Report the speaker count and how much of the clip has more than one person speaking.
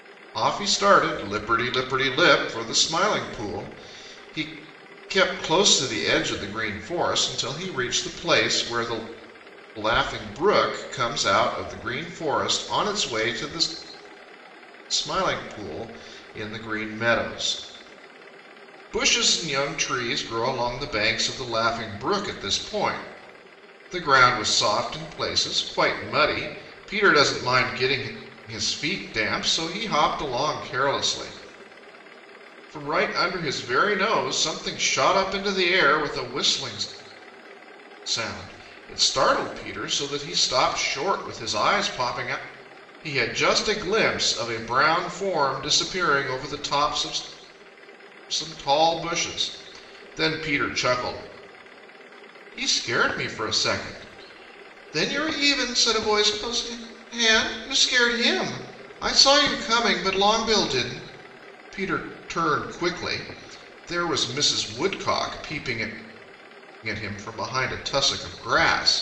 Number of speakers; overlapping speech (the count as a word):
one, no overlap